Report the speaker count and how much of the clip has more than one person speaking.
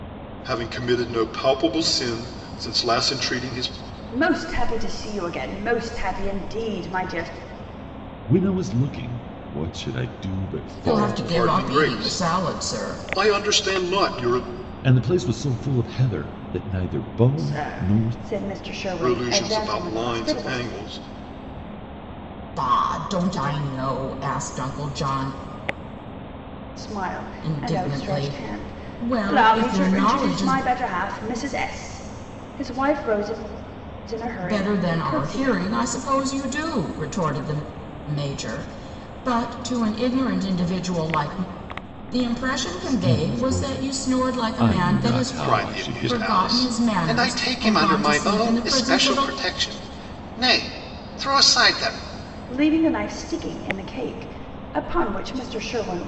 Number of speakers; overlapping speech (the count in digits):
4, about 28%